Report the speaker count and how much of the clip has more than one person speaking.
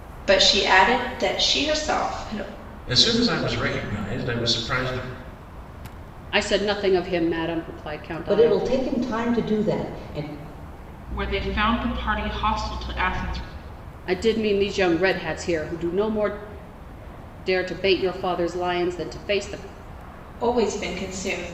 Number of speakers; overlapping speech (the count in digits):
5, about 2%